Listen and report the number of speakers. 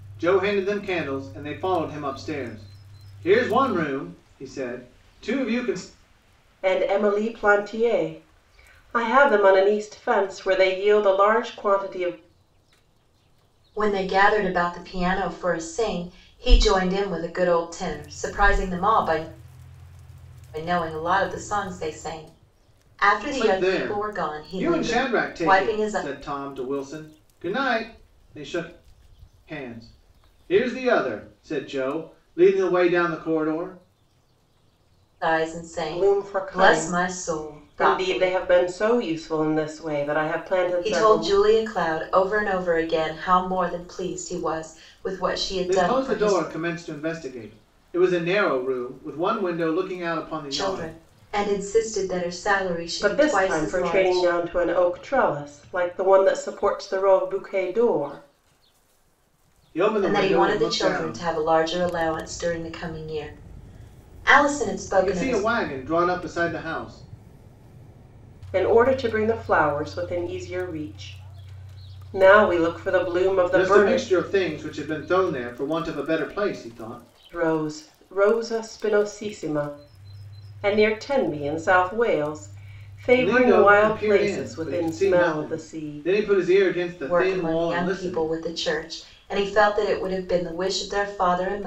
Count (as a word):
three